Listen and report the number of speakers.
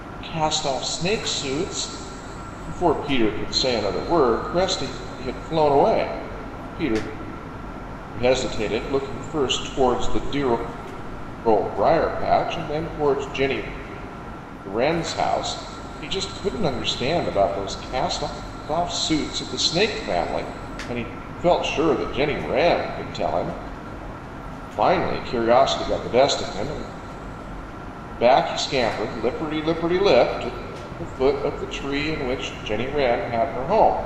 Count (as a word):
one